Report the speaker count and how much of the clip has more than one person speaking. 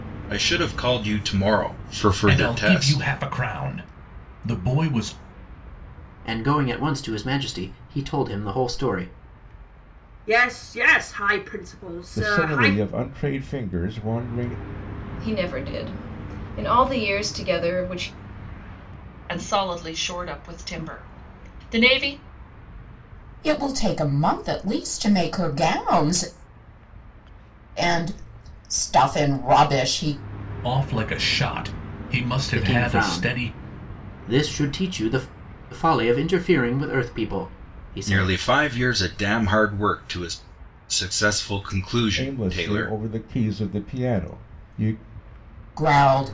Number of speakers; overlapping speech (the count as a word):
eight, about 8%